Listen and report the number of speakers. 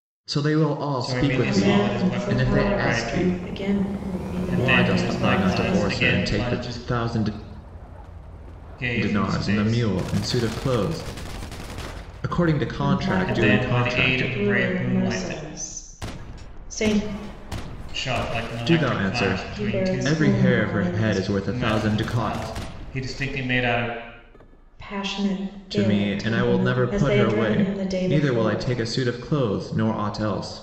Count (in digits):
3